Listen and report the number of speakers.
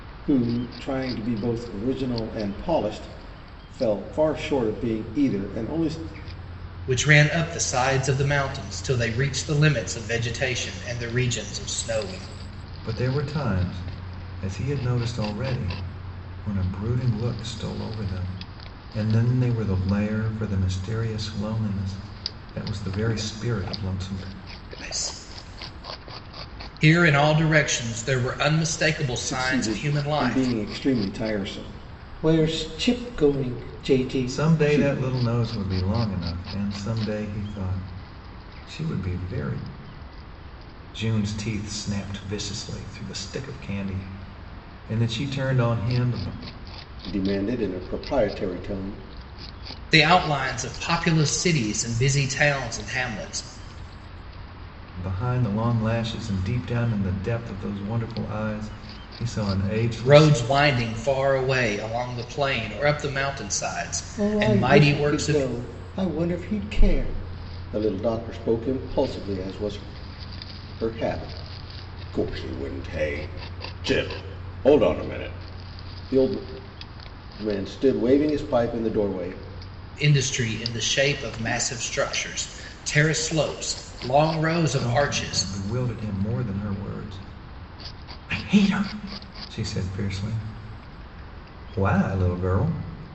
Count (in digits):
3